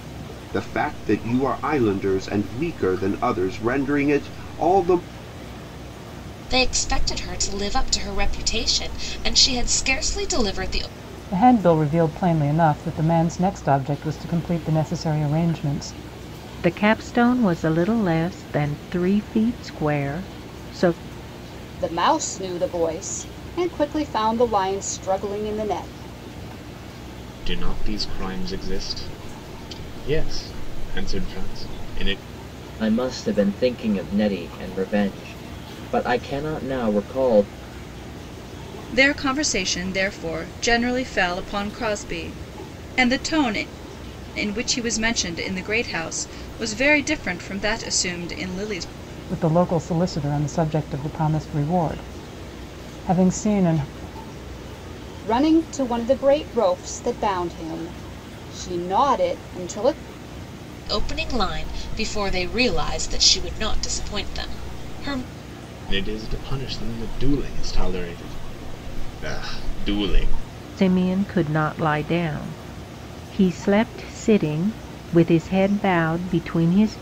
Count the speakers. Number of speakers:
eight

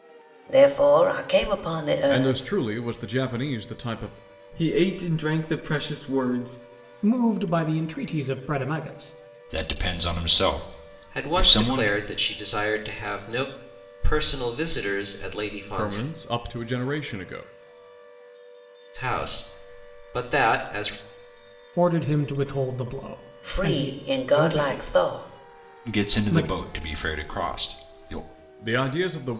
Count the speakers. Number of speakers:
six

